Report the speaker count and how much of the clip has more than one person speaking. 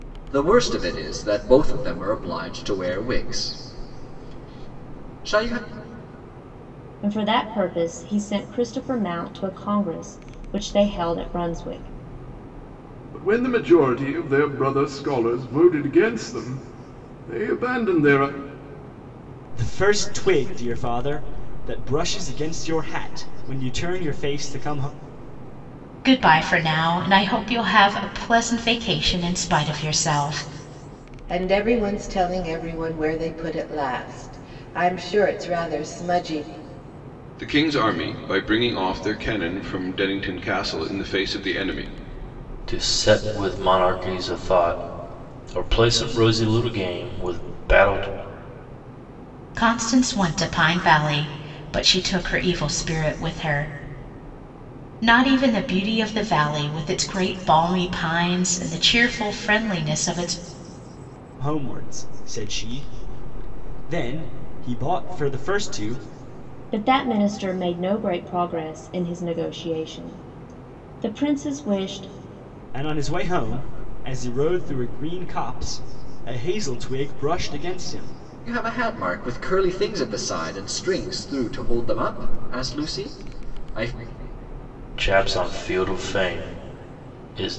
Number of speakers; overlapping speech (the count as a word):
eight, no overlap